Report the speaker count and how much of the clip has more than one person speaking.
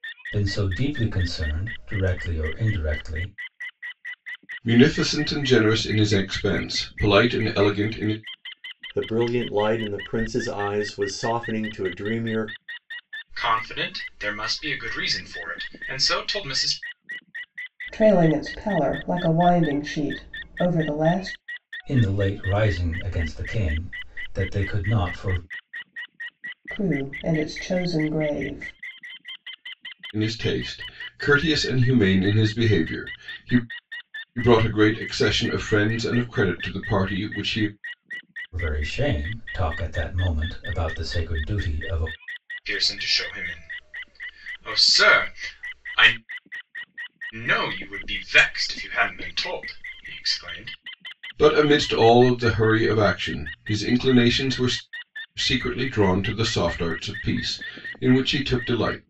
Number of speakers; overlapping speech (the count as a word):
five, no overlap